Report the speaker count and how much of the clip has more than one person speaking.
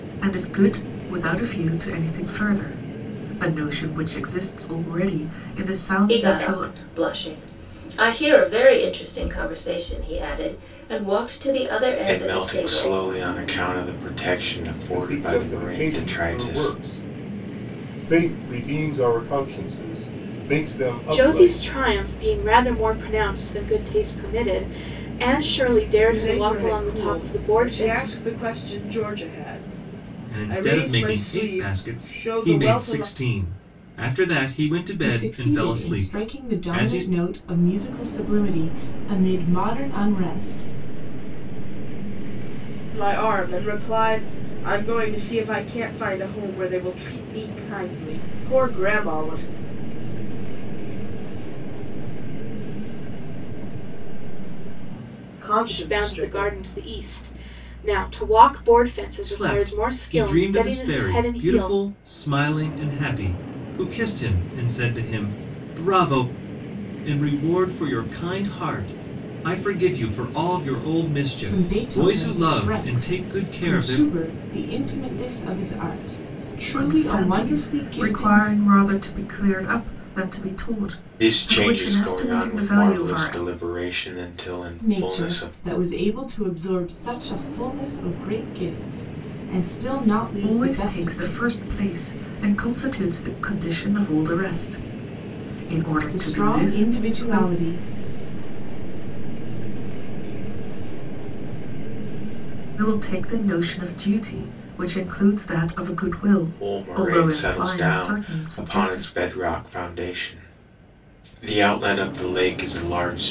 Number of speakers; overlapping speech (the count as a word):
nine, about 31%